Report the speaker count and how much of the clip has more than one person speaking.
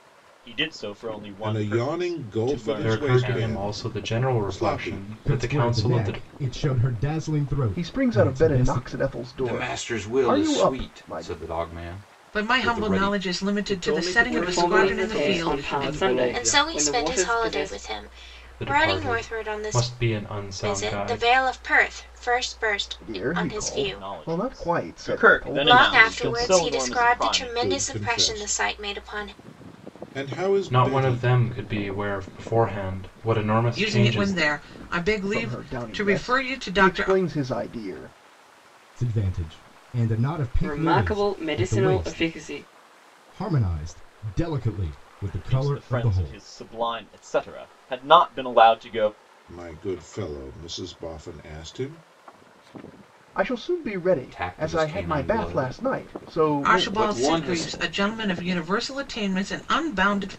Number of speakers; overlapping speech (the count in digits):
10, about 51%